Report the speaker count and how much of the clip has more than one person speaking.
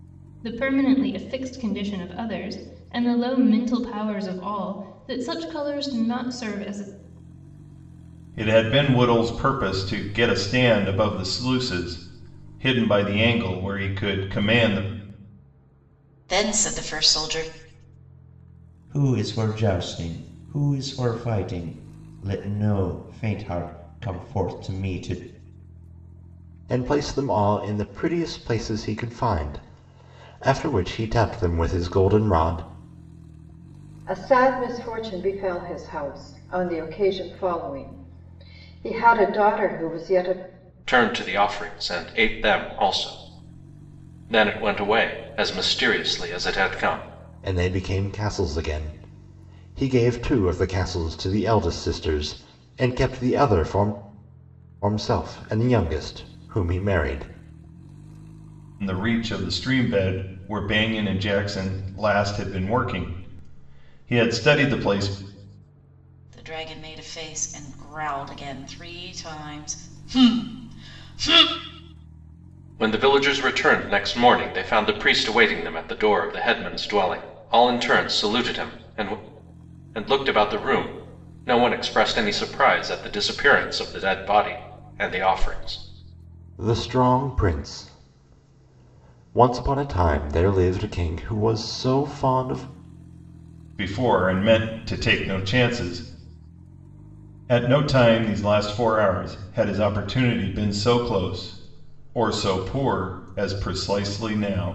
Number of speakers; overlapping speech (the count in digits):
7, no overlap